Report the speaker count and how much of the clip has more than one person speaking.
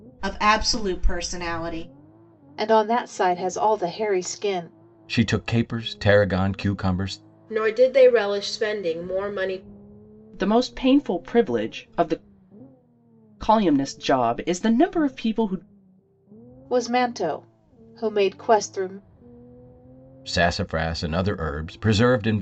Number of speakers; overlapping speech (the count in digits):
5, no overlap